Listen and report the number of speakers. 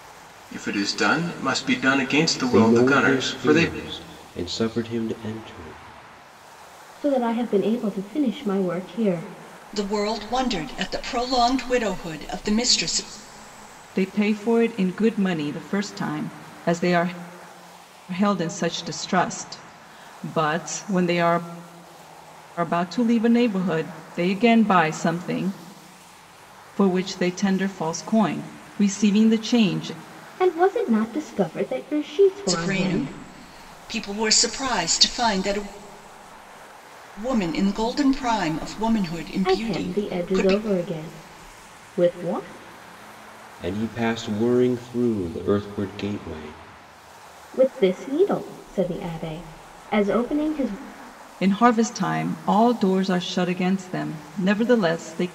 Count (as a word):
five